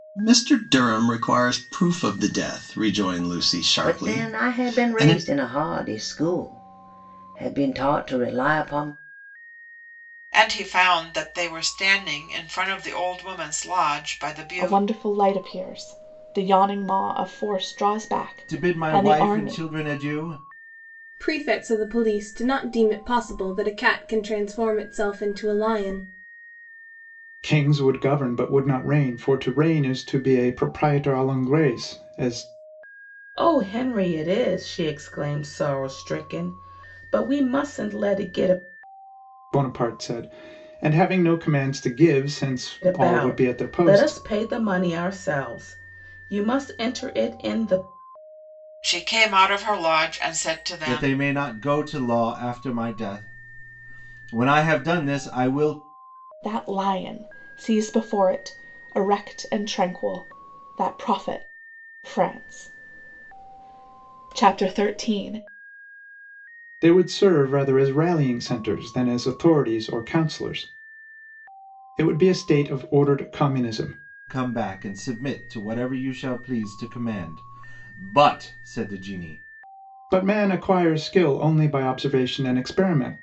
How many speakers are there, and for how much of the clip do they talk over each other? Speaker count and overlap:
eight, about 6%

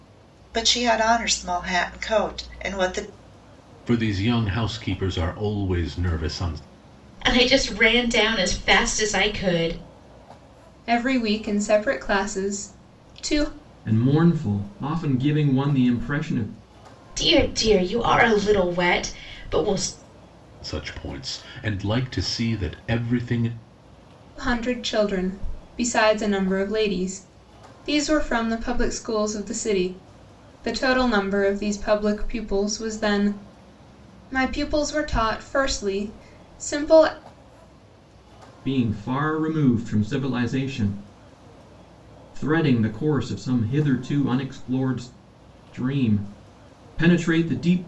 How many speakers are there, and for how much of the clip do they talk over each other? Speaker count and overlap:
five, no overlap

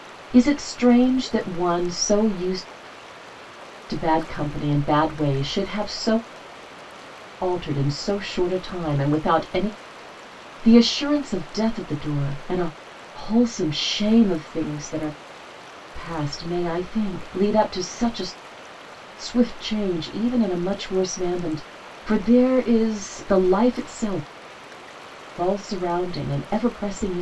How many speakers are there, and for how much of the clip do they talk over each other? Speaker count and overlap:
one, no overlap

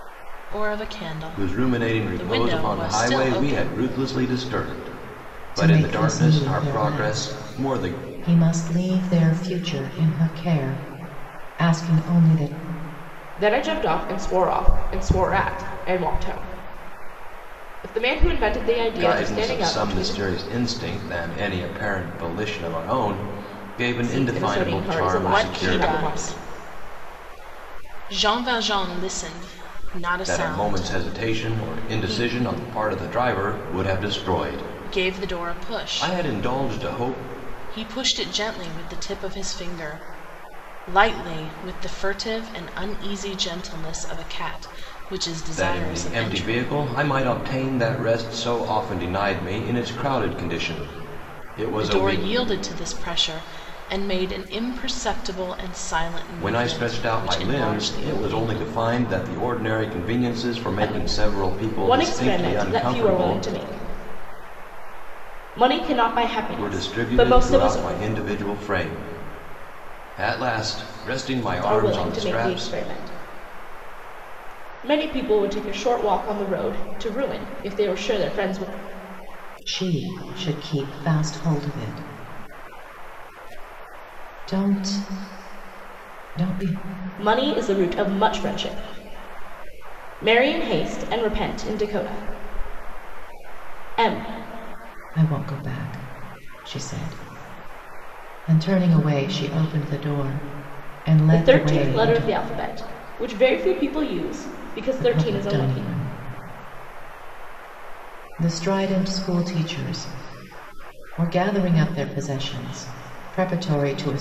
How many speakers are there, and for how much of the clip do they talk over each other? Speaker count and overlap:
four, about 22%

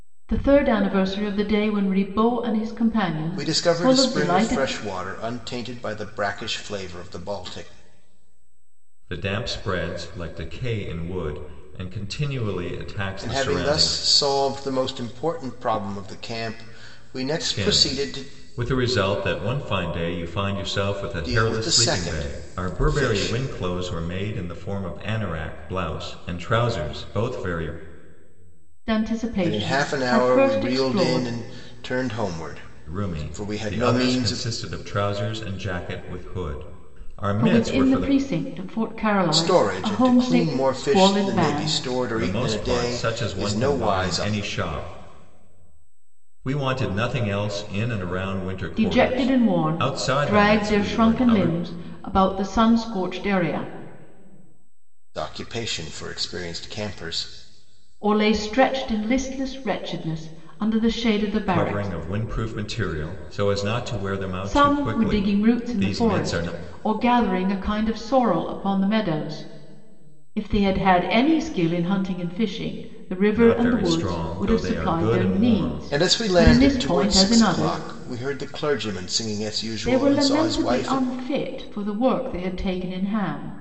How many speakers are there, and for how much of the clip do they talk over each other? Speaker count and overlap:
three, about 31%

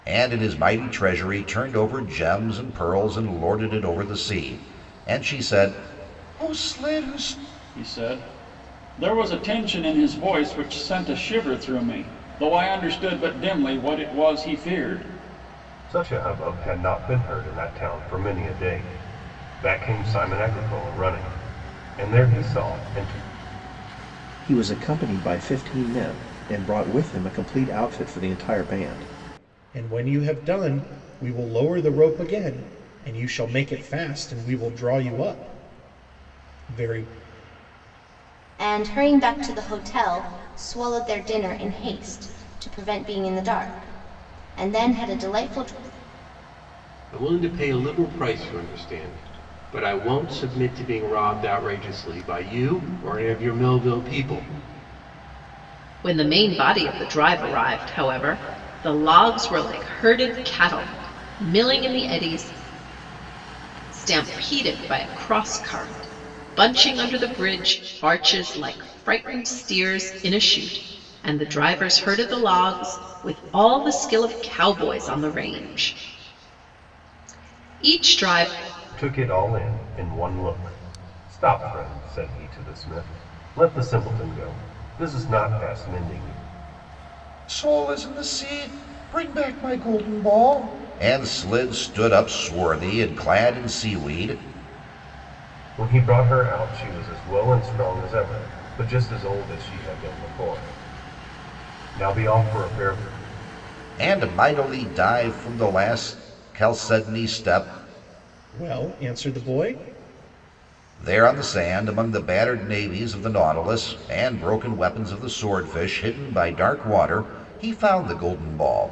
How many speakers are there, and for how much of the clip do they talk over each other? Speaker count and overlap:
eight, no overlap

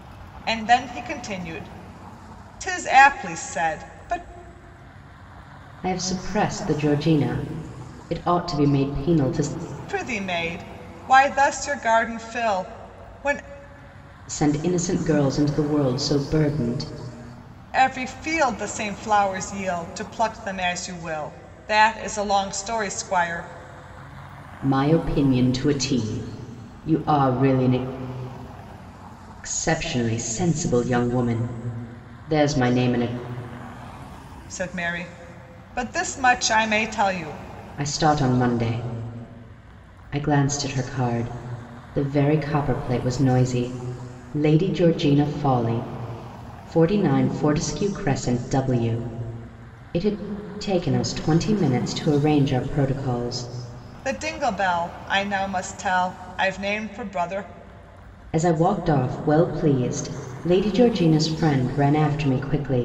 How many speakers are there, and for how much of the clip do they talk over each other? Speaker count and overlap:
two, no overlap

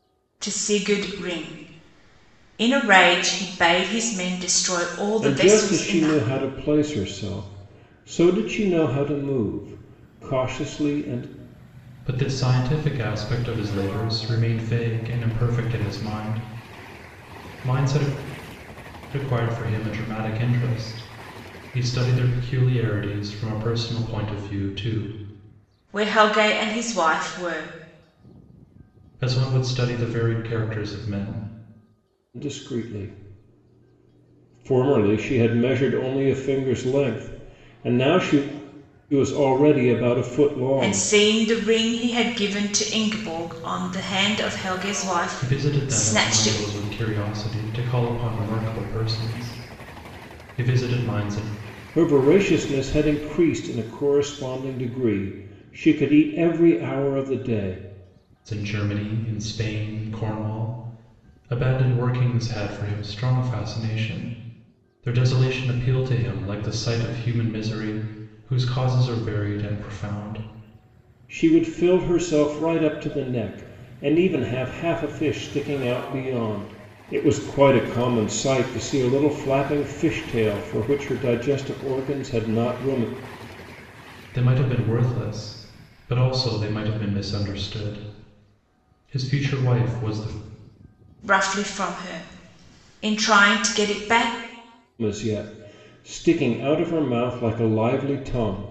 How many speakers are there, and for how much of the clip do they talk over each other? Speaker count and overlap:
three, about 3%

